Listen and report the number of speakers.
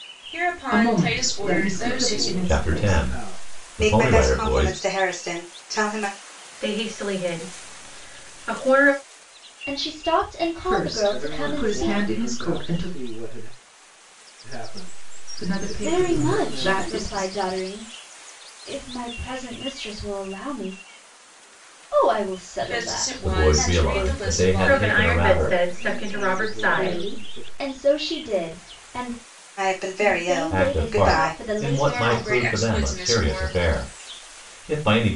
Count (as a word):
seven